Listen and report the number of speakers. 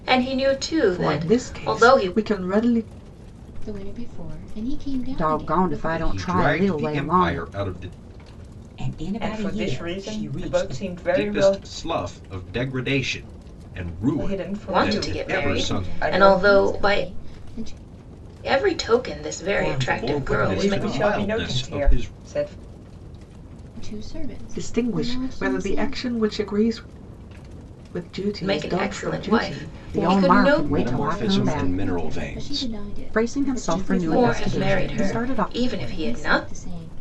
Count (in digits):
7